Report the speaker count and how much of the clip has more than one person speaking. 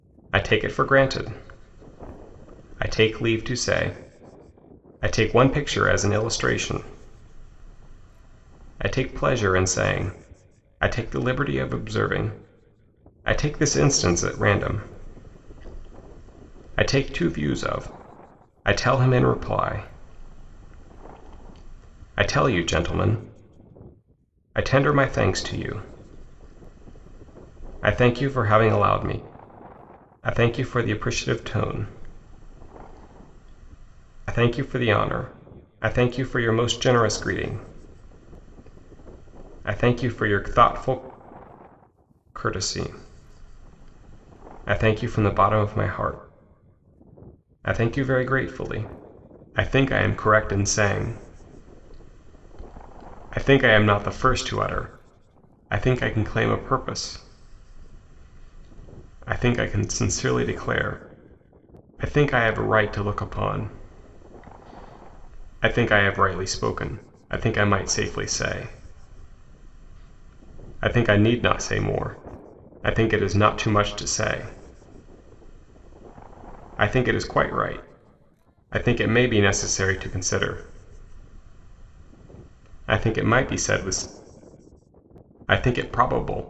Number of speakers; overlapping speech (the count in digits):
1, no overlap